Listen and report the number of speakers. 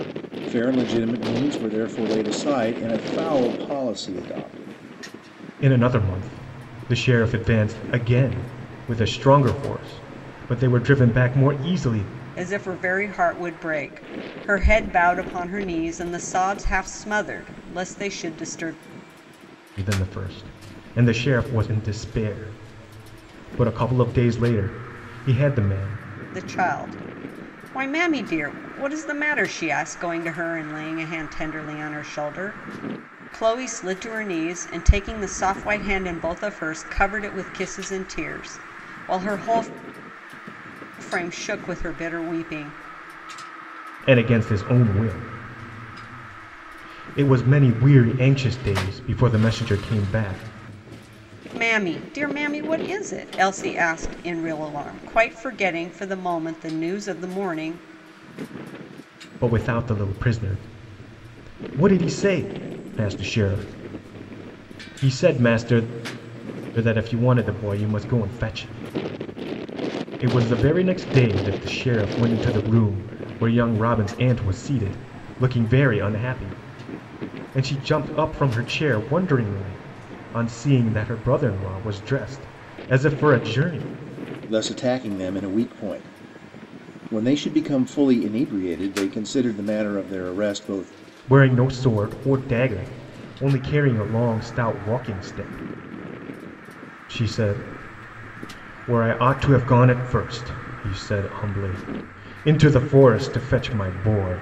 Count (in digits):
3